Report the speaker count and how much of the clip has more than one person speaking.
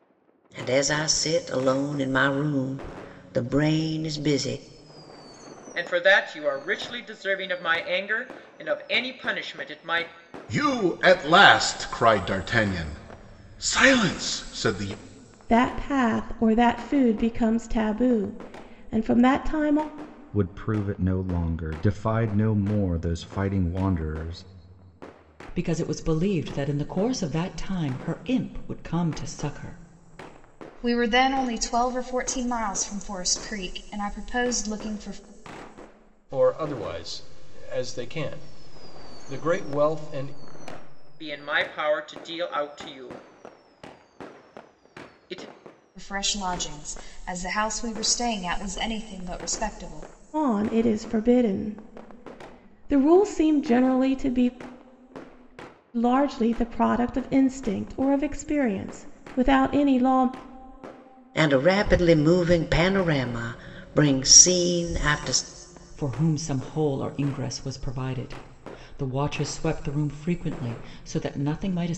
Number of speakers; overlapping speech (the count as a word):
eight, no overlap